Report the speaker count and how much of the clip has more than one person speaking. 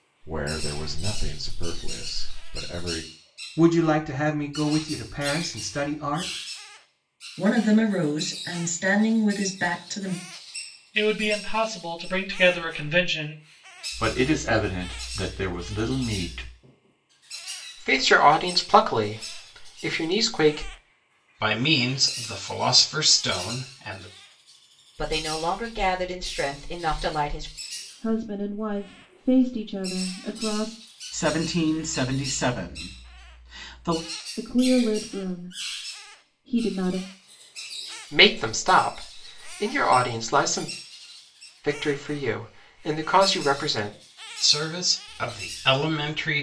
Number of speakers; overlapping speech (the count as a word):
ten, no overlap